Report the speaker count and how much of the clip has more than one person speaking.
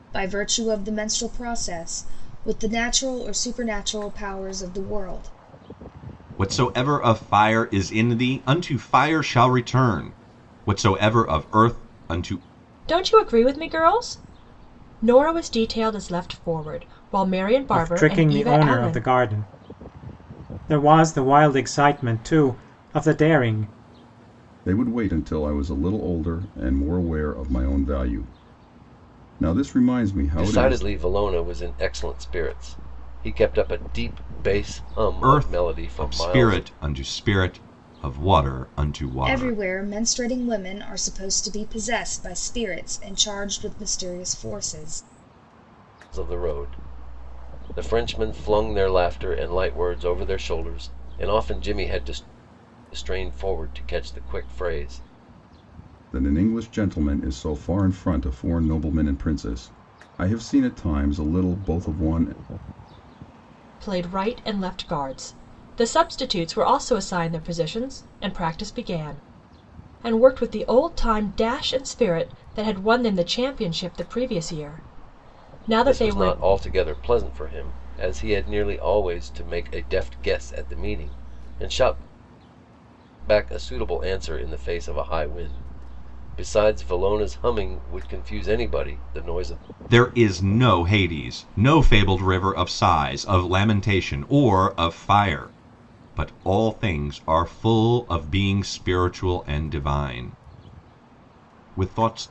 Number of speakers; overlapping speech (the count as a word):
six, about 4%